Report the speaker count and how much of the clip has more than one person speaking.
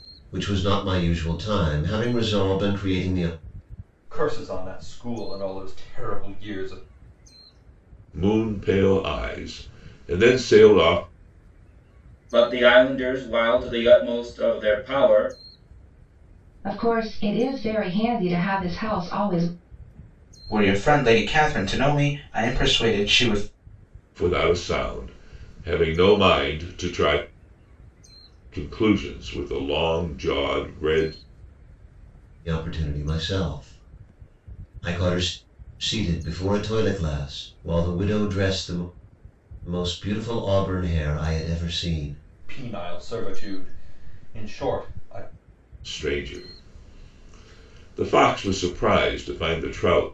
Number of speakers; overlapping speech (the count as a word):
six, no overlap